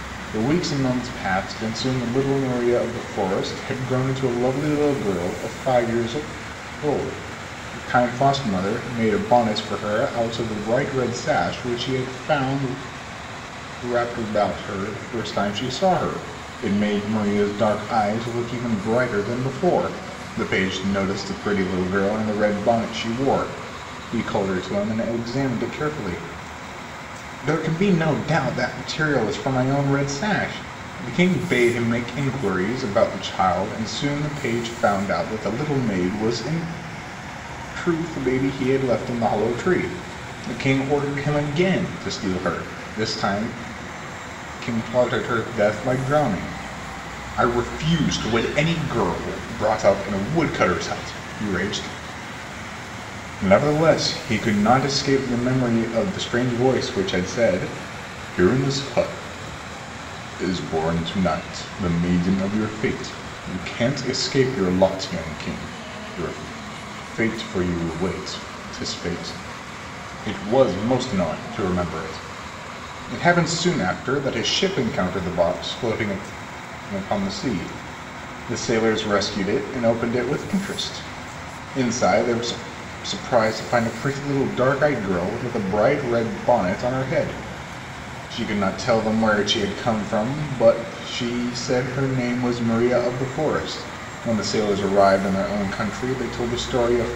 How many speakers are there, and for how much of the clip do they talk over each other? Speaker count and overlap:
1, no overlap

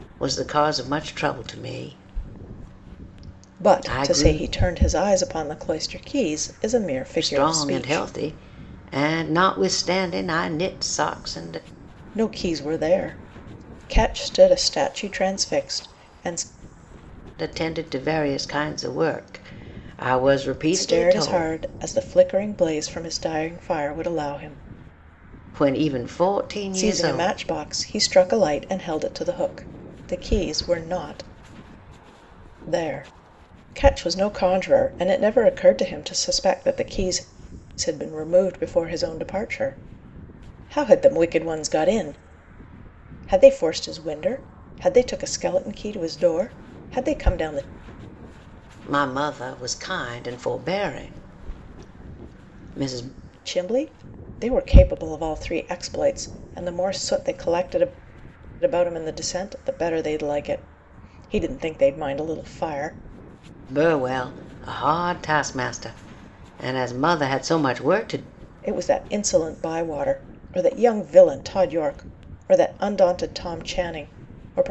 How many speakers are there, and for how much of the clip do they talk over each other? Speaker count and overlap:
2, about 5%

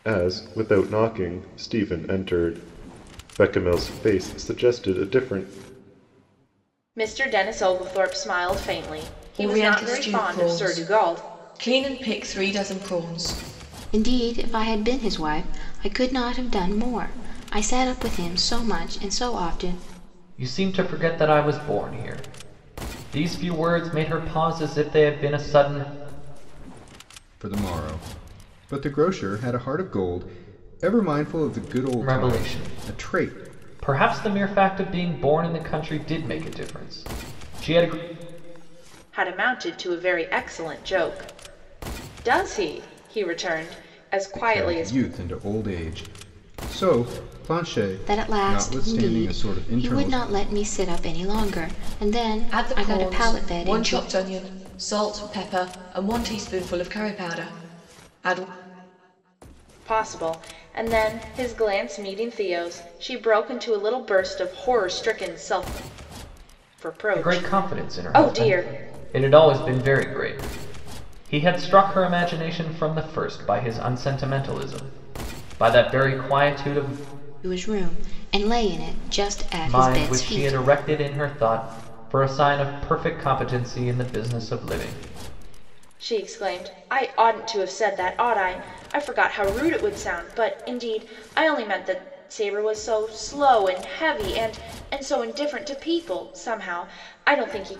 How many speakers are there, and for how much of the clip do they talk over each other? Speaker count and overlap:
6, about 10%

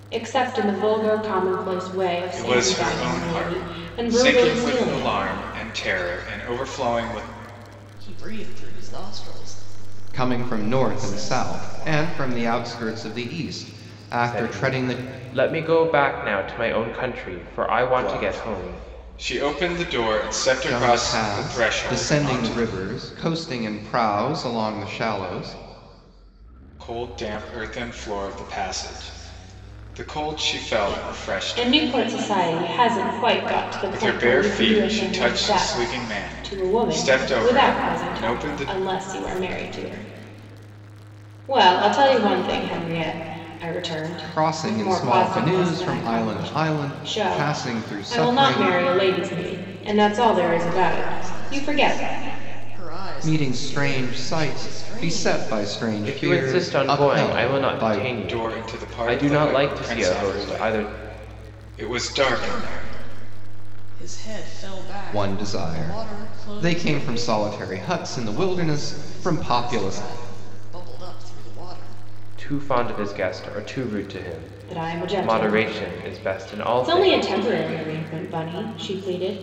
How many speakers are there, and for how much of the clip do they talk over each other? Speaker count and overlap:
5, about 44%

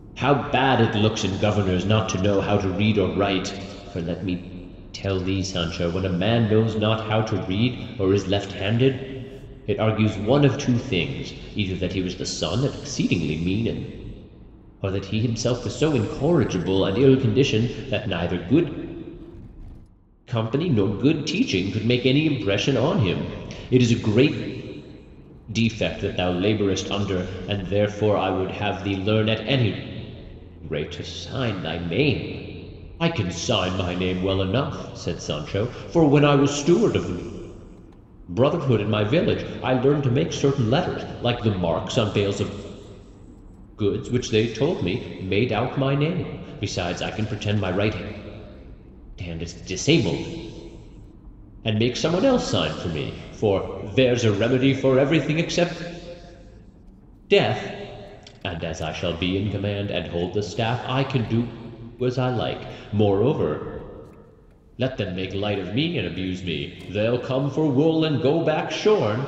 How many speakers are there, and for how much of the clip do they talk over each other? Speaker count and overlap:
1, no overlap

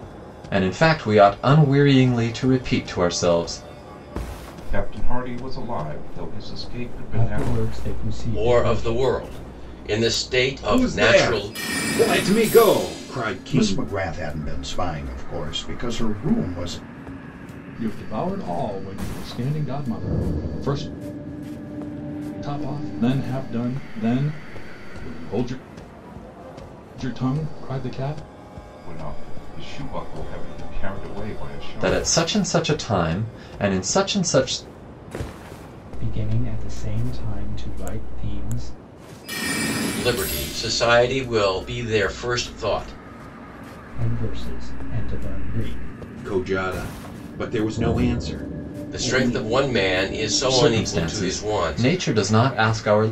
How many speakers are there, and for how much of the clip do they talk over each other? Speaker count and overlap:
7, about 9%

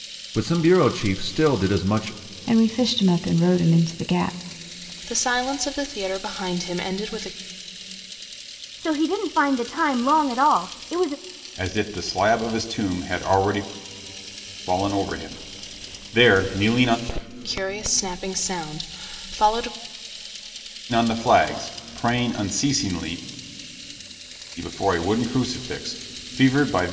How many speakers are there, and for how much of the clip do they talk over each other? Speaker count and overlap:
5, no overlap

